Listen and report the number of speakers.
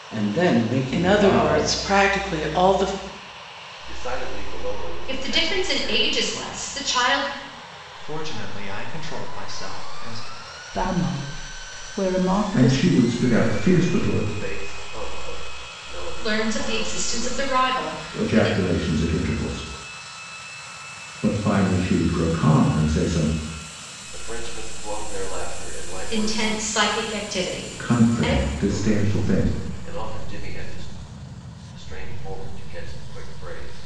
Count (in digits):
7